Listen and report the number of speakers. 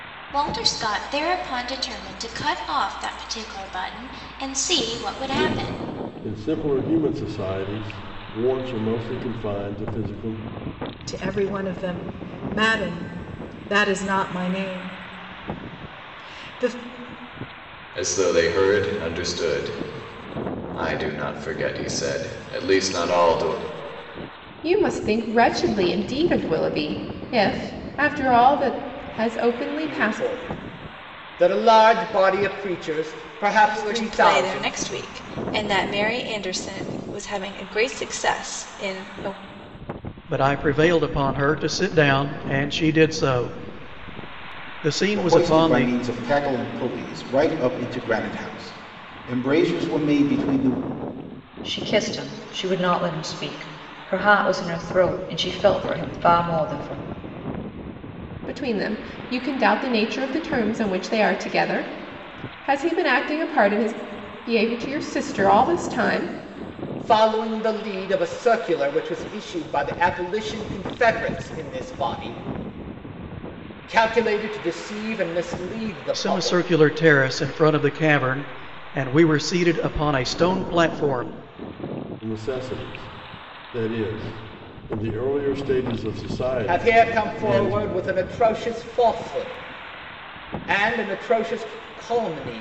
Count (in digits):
10